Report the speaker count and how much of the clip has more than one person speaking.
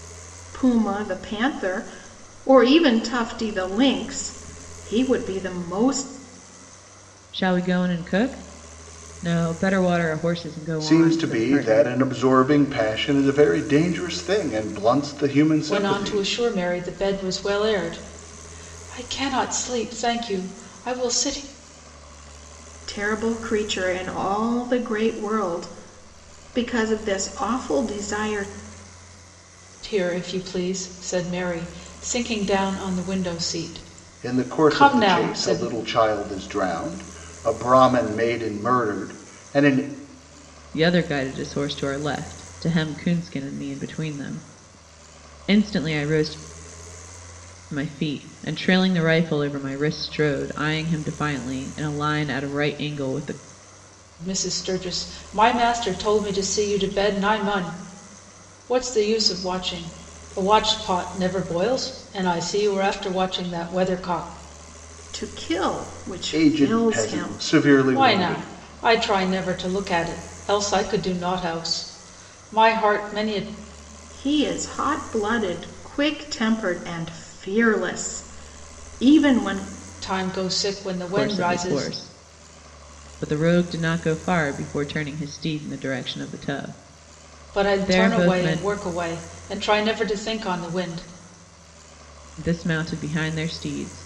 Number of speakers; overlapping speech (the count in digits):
4, about 8%